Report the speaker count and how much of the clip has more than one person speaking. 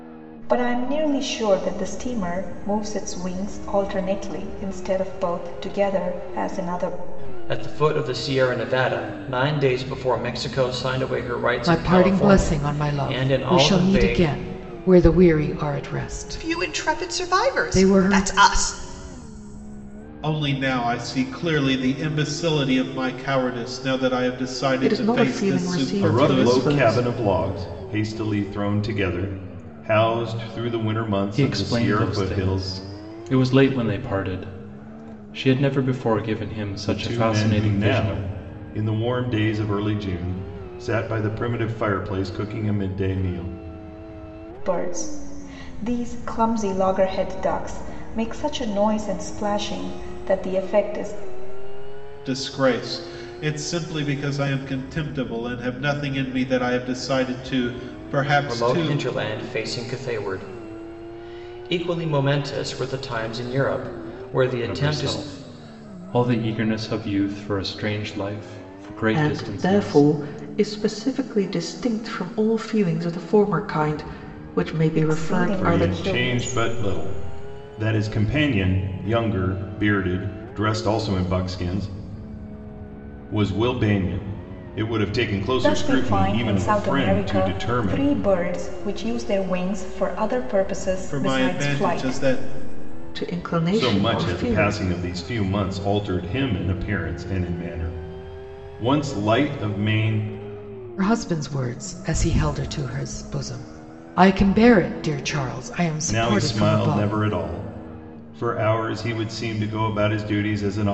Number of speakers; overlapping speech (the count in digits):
8, about 18%